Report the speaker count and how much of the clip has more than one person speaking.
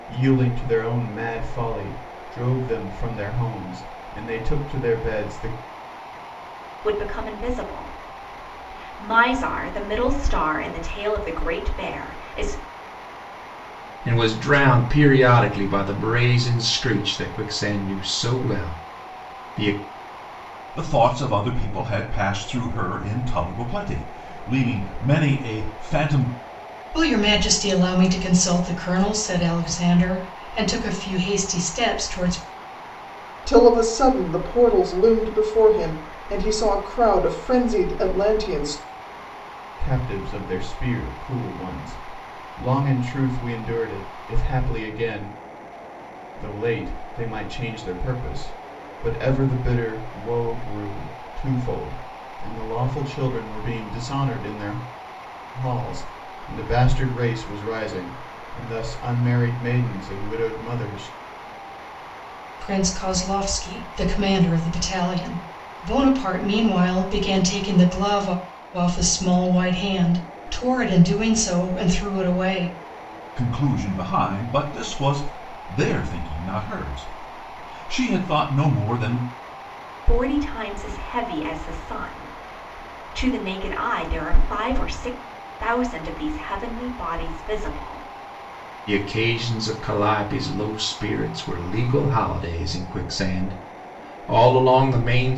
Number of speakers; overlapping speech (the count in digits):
6, no overlap